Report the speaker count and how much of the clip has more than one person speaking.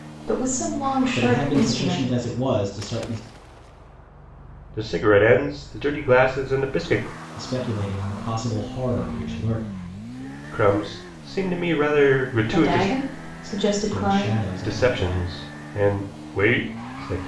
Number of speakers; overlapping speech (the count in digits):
3, about 17%